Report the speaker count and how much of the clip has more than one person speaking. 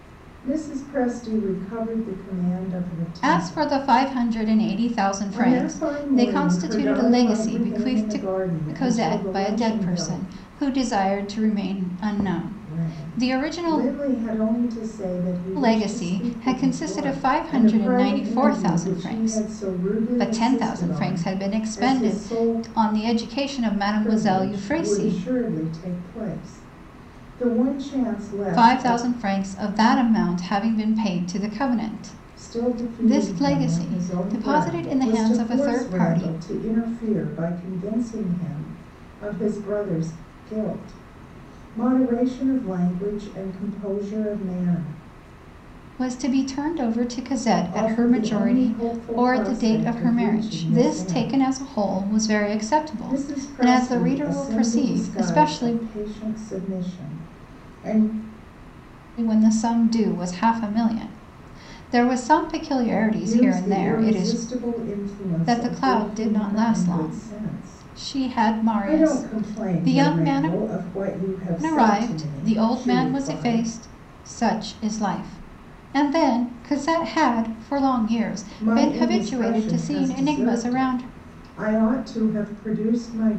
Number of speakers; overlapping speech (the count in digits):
2, about 42%